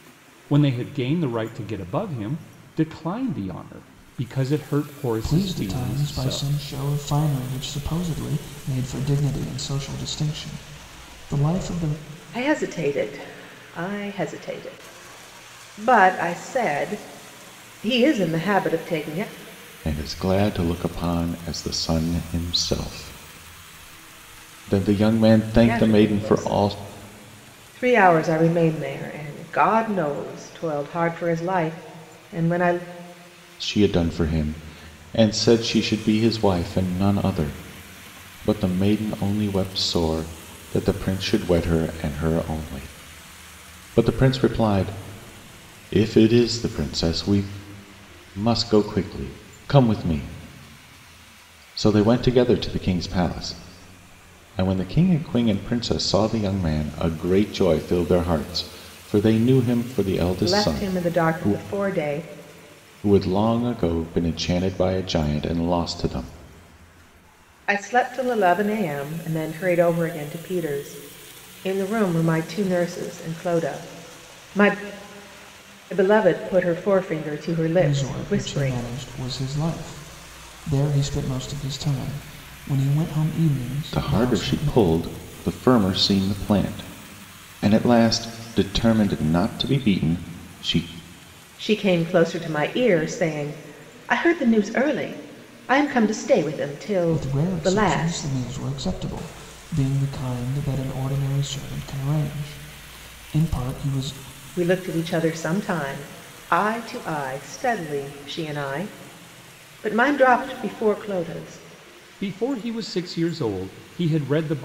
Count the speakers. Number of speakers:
four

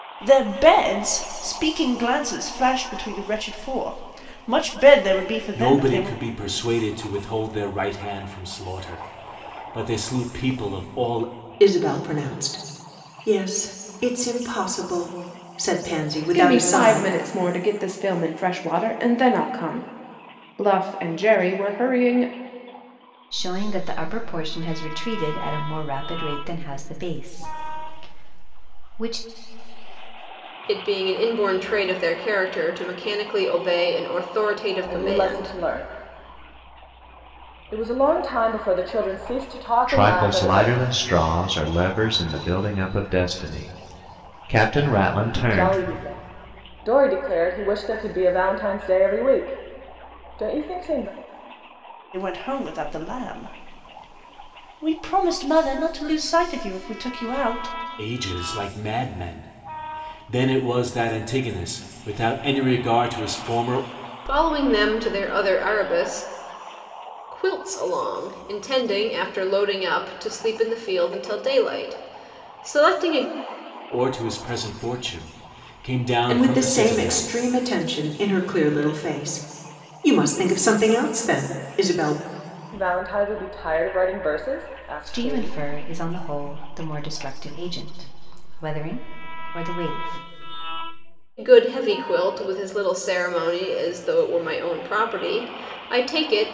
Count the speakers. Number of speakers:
eight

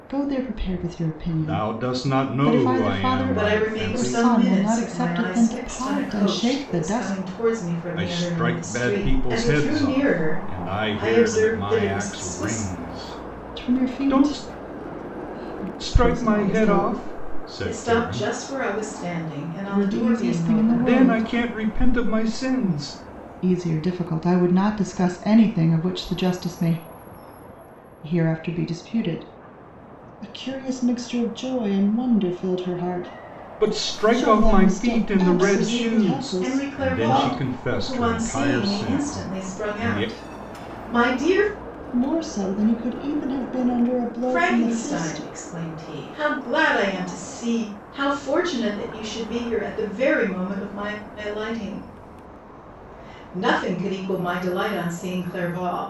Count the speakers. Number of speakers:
three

